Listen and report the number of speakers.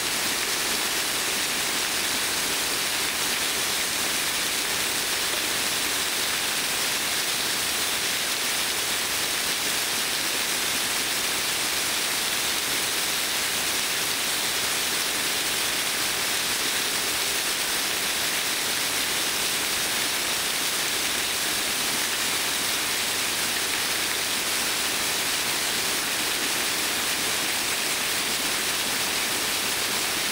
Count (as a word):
zero